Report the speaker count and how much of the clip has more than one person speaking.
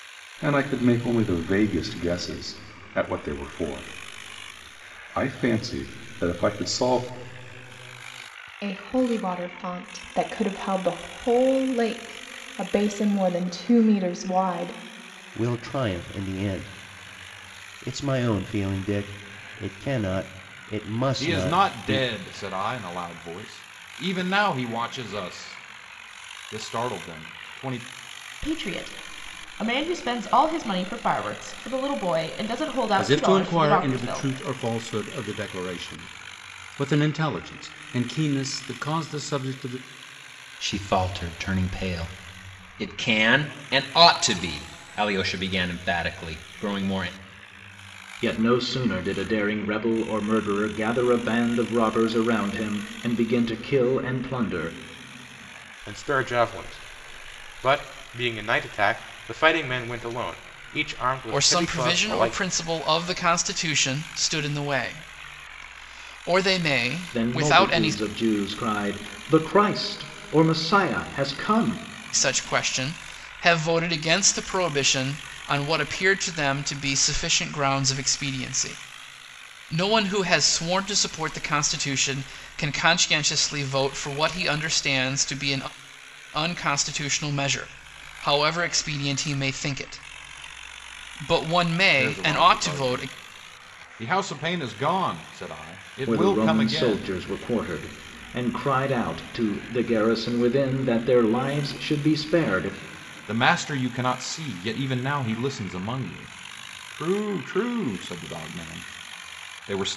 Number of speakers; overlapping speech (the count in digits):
10, about 6%